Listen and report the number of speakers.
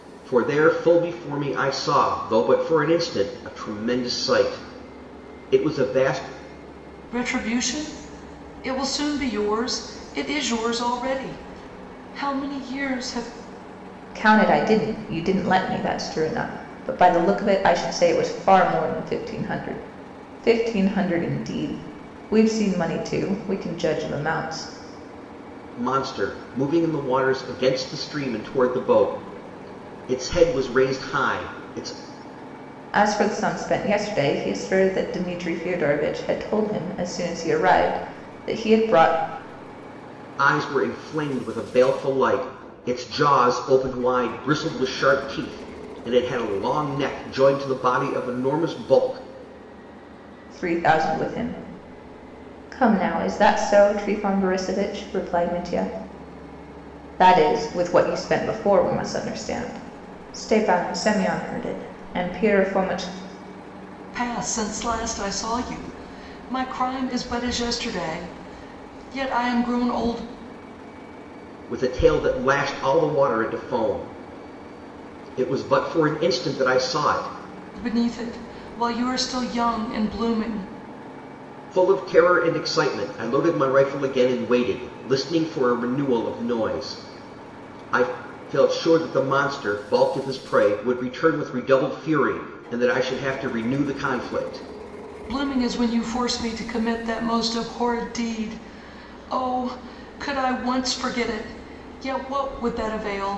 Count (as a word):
three